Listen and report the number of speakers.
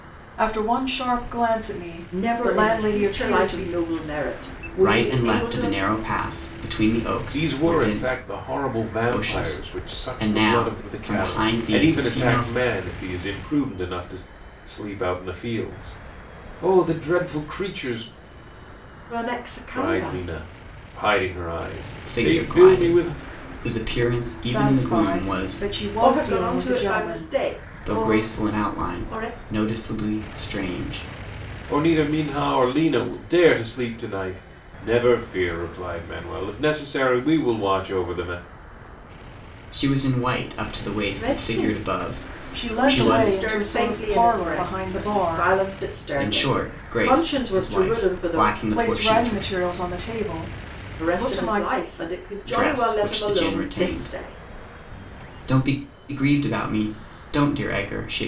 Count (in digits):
4